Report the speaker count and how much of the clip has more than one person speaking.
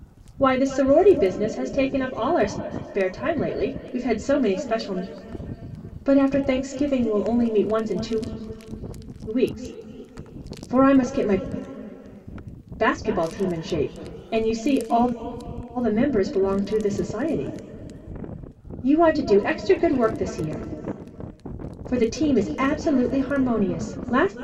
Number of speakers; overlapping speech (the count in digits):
1, no overlap